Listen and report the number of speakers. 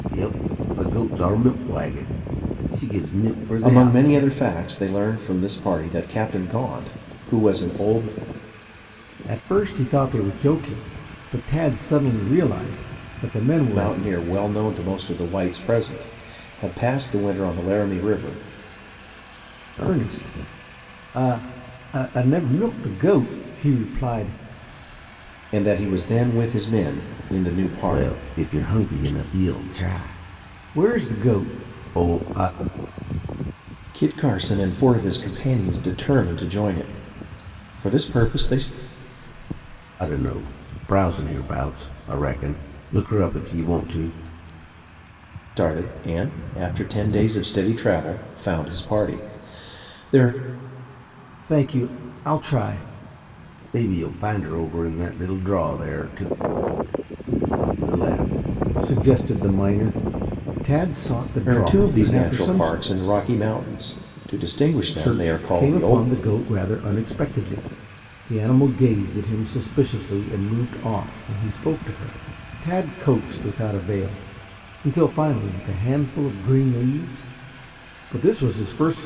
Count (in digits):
2